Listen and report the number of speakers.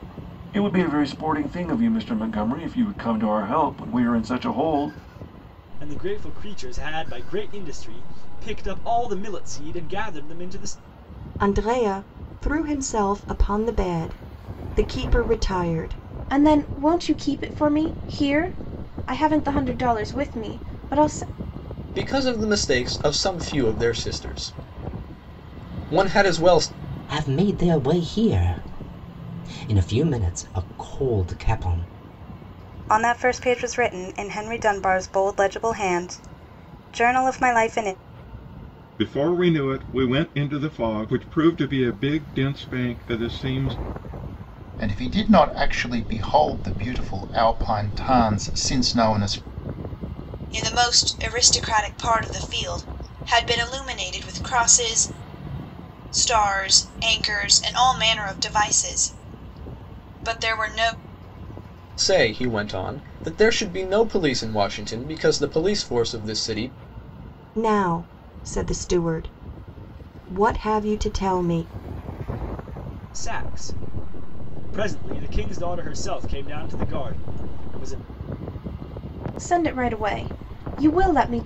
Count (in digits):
10